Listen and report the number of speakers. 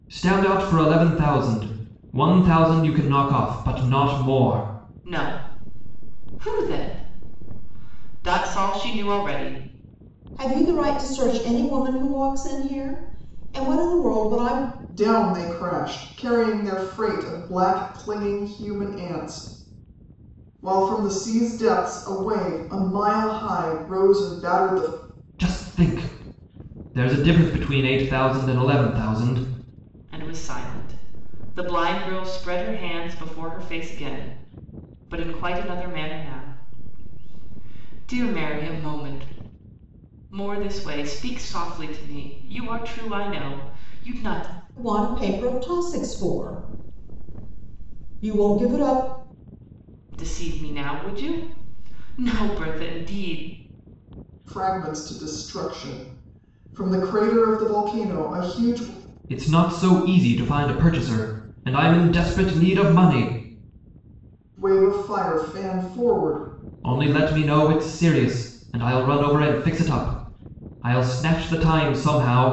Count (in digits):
4